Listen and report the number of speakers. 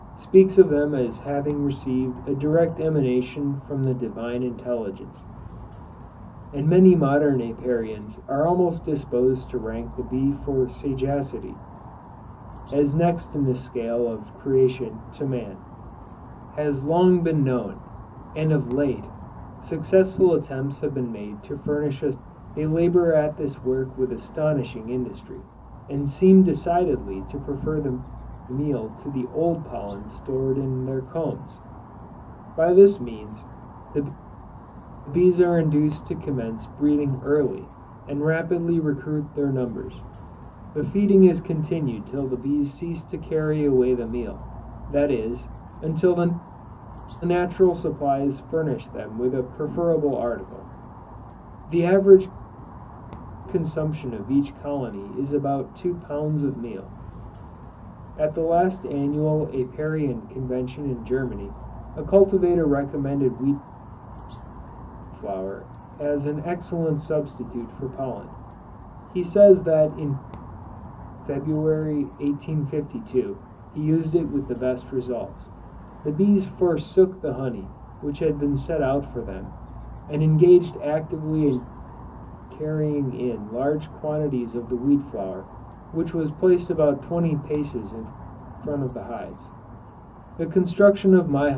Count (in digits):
1